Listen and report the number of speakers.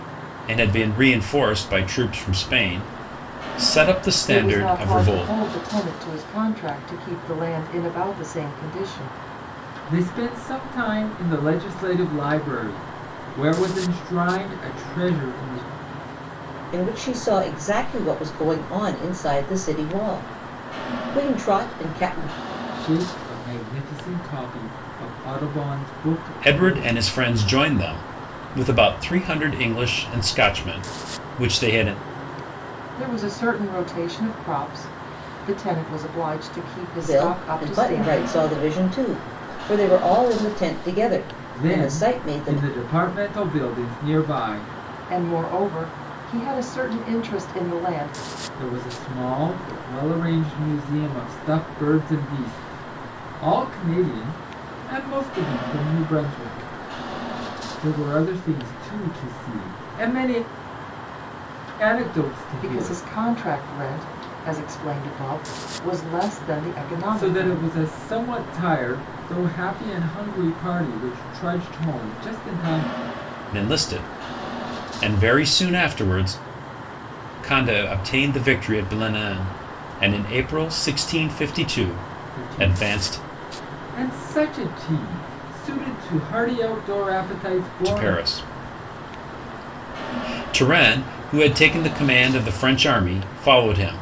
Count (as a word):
four